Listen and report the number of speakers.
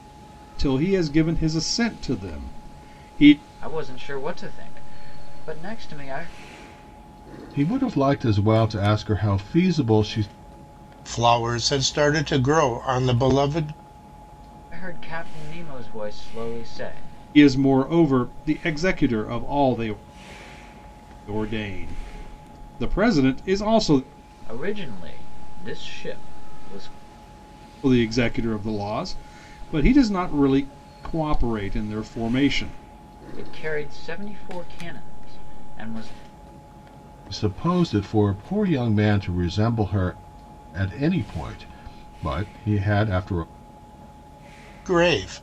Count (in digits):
4